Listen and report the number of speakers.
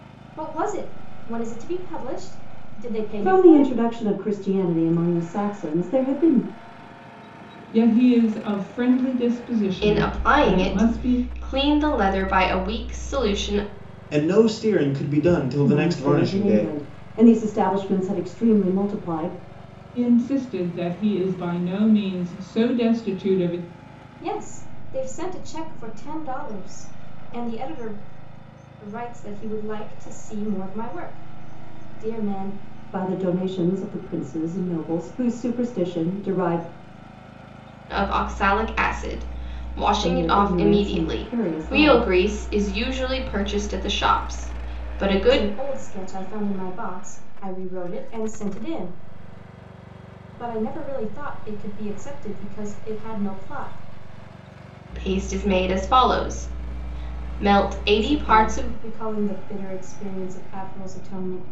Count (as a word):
five